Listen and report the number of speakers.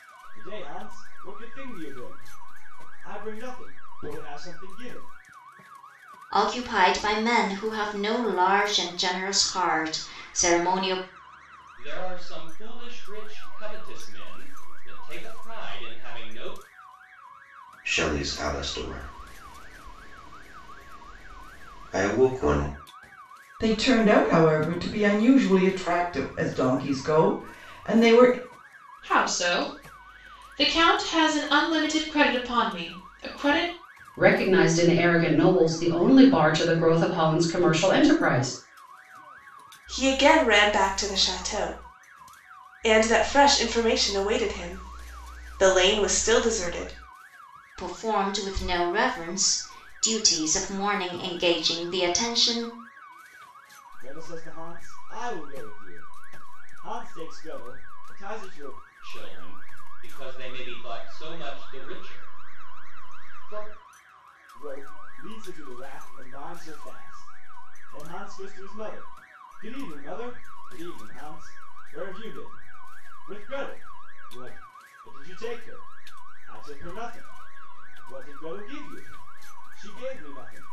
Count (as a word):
eight